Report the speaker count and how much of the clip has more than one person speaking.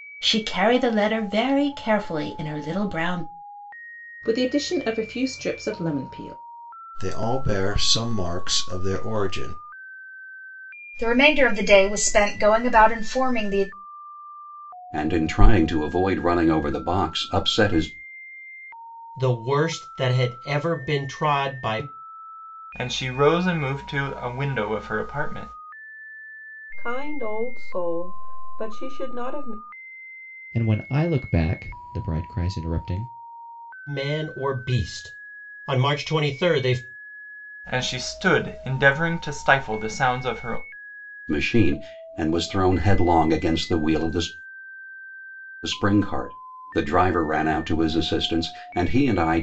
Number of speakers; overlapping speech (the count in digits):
9, no overlap